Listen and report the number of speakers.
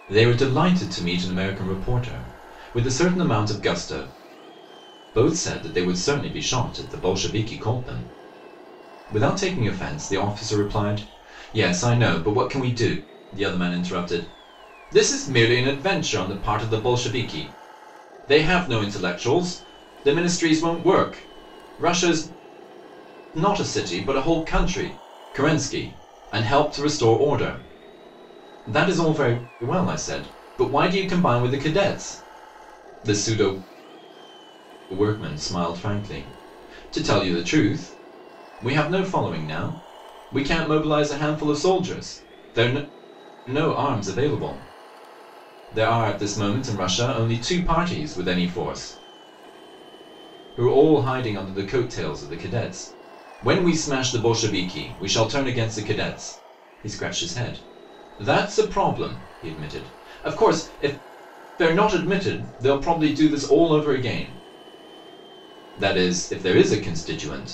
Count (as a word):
one